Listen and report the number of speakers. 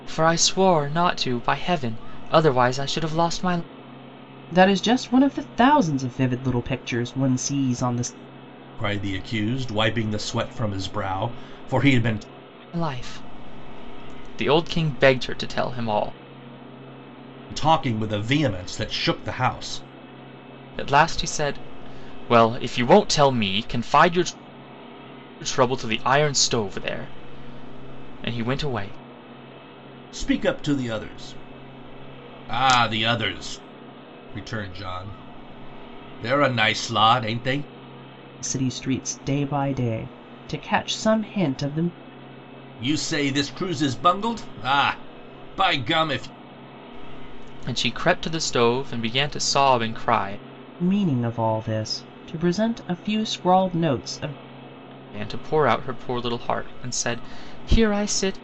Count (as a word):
three